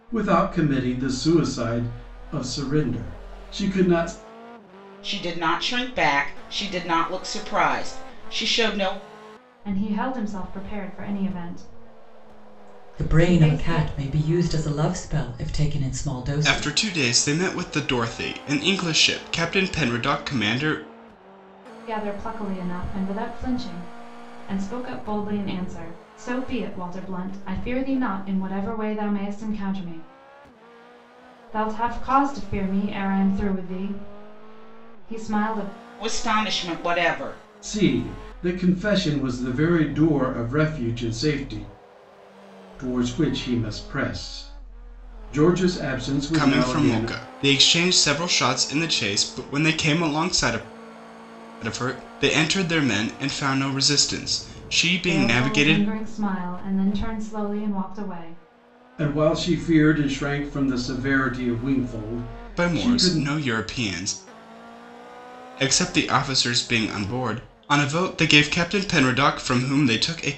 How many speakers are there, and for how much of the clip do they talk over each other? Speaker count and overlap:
five, about 5%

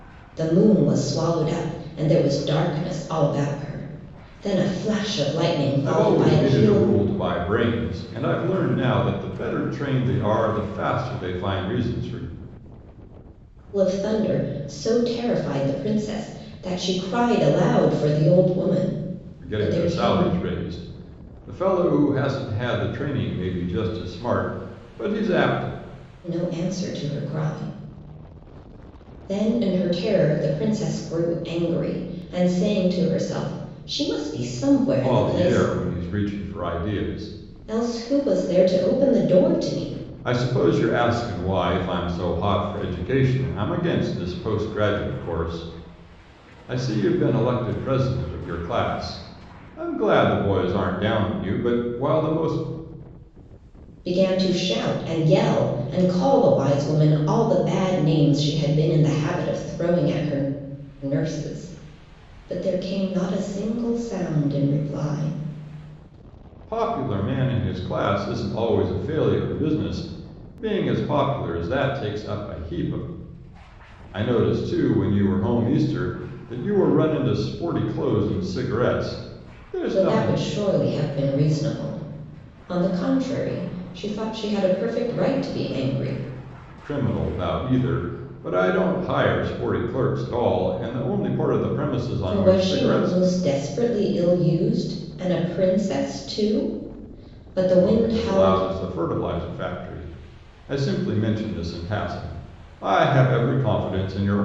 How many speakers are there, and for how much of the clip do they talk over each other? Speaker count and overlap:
two, about 5%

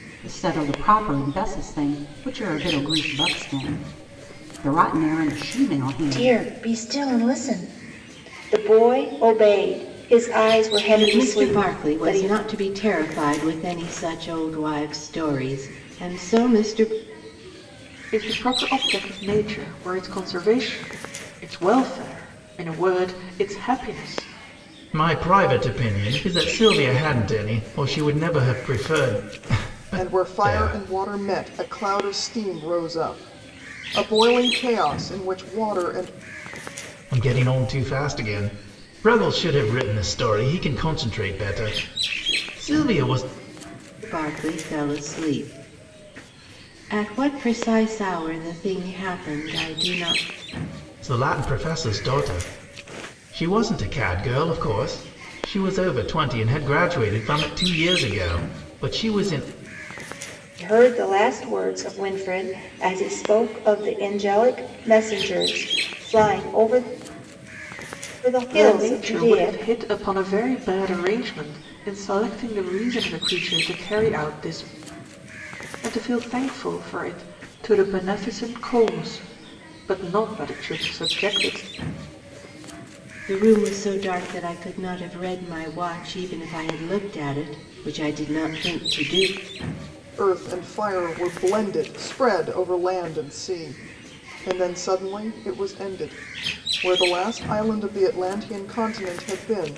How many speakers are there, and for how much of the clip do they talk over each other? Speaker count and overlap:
six, about 4%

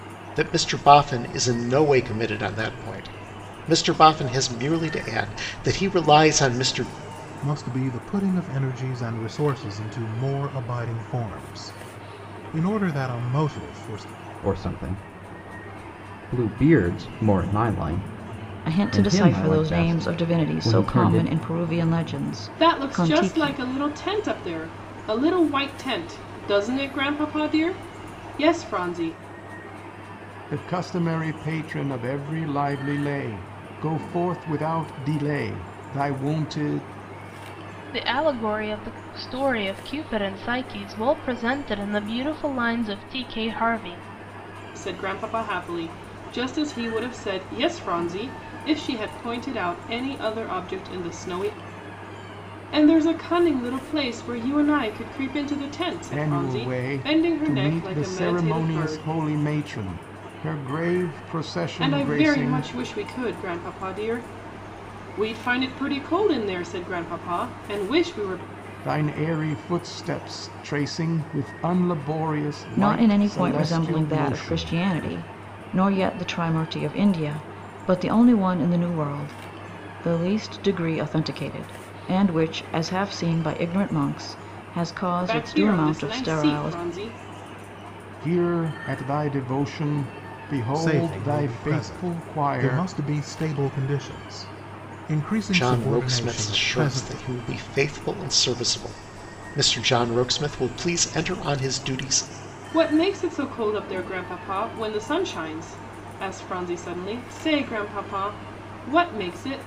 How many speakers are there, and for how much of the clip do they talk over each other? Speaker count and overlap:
seven, about 14%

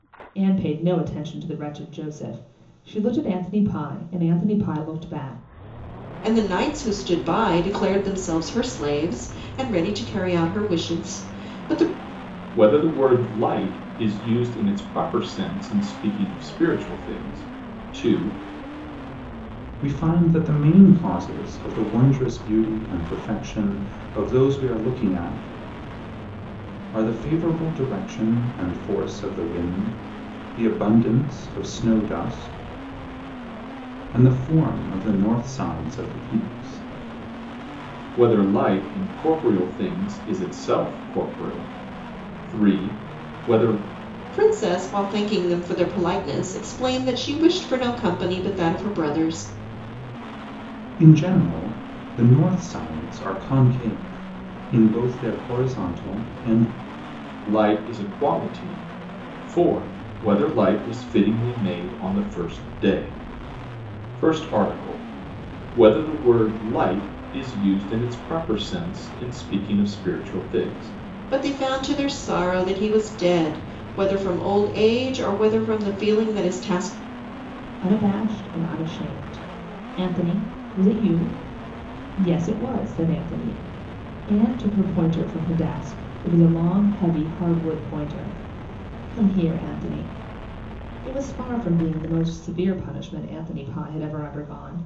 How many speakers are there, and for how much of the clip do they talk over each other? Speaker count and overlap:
four, no overlap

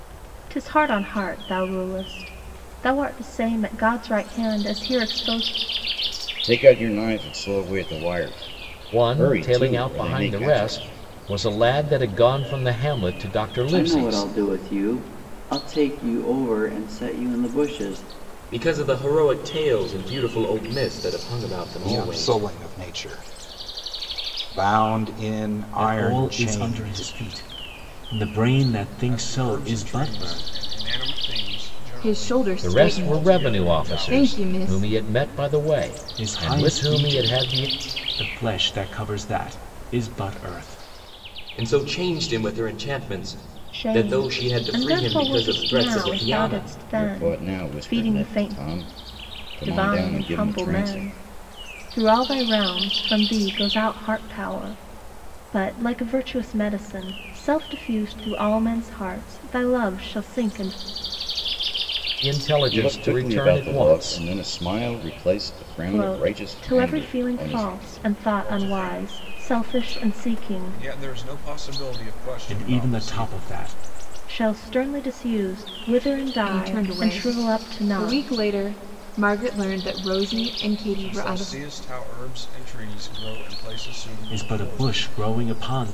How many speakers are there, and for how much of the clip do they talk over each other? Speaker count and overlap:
nine, about 32%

